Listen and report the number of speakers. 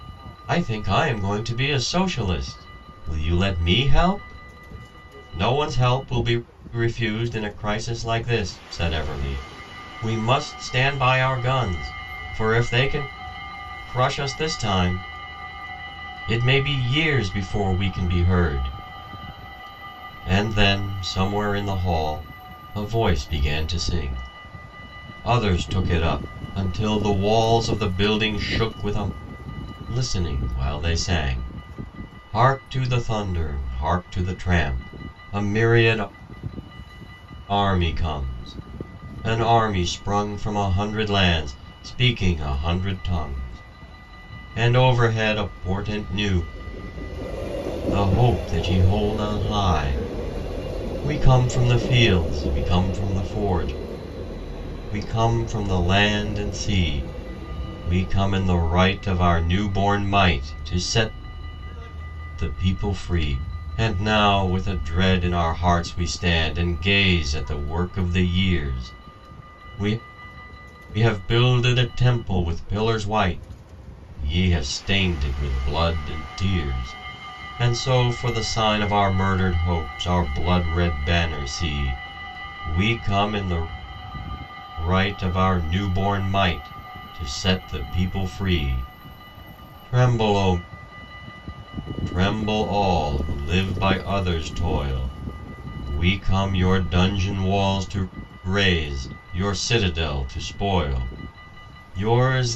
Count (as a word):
one